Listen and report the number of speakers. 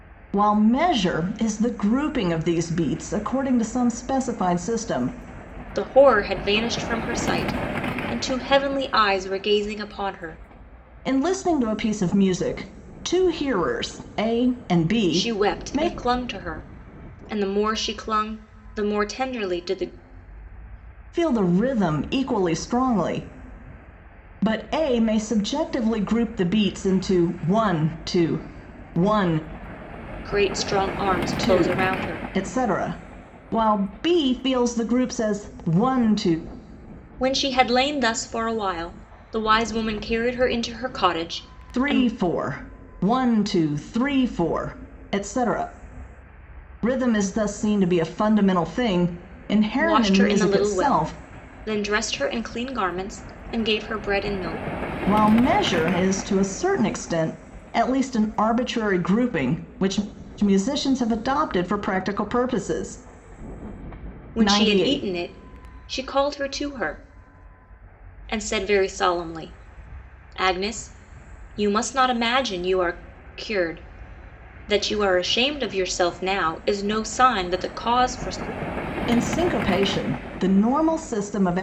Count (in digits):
2